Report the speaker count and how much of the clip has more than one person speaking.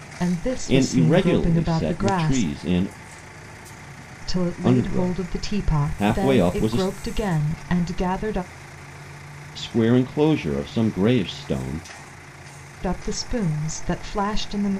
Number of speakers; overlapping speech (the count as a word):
two, about 28%